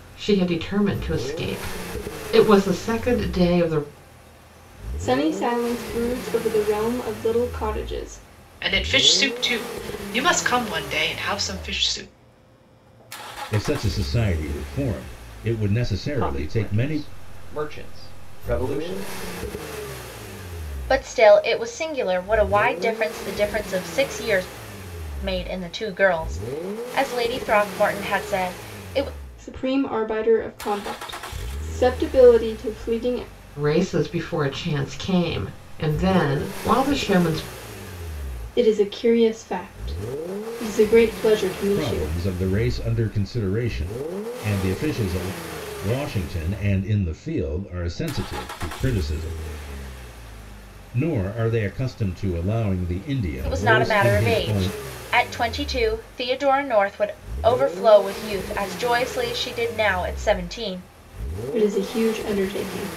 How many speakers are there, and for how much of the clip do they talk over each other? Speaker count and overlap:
six, about 4%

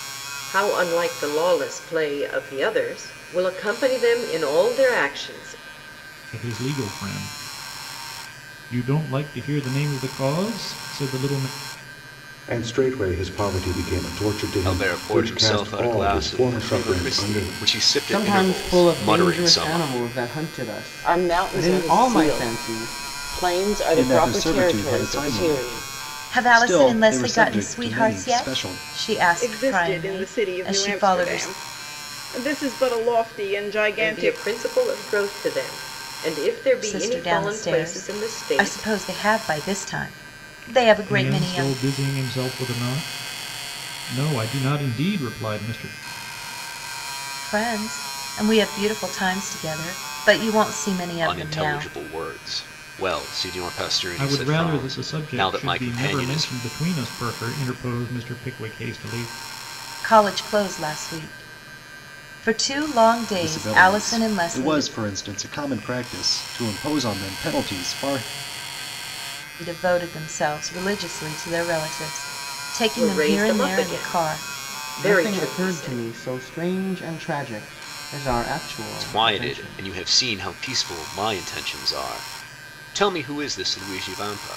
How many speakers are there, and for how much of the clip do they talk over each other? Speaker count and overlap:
nine, about 29%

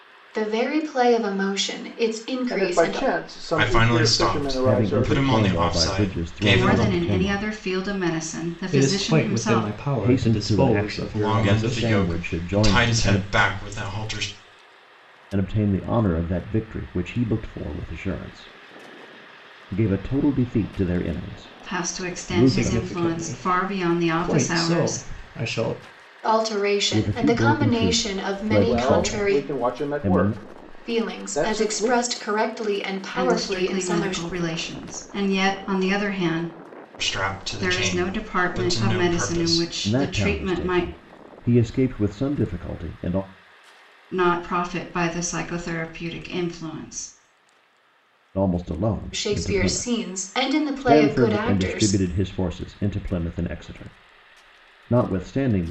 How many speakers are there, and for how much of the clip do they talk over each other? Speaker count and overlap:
six, about 44%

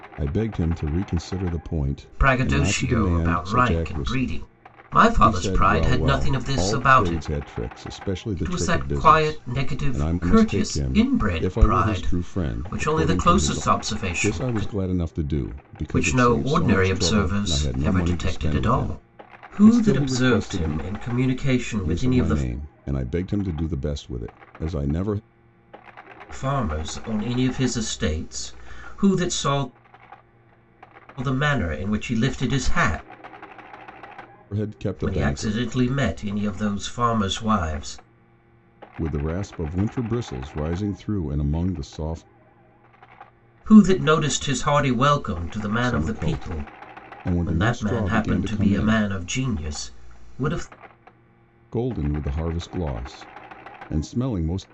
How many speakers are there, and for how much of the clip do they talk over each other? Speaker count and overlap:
two, about 35%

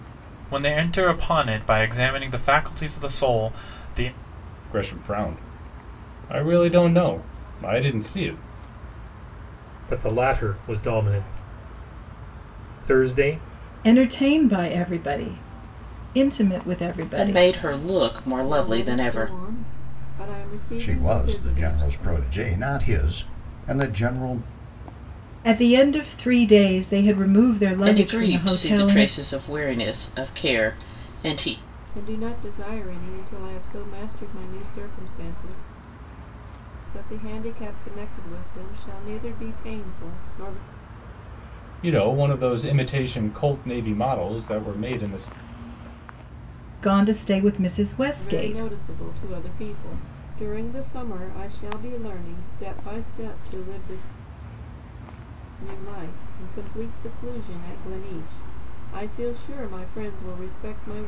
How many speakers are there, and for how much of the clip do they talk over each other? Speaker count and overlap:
seven, about 7%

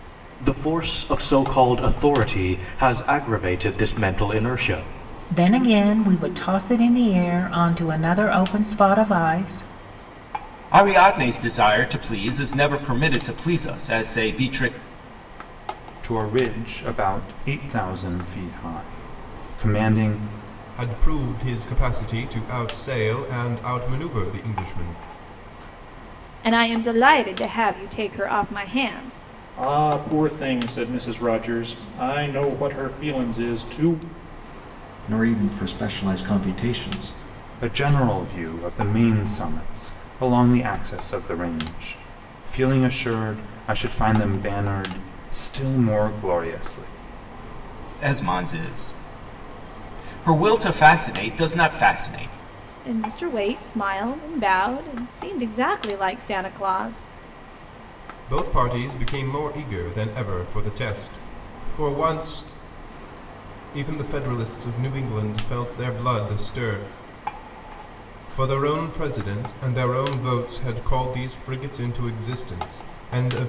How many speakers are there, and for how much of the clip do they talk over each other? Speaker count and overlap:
eight, no overlap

